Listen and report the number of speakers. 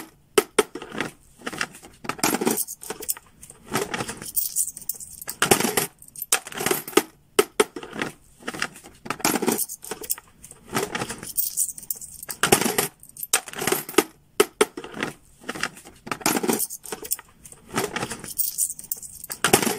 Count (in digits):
0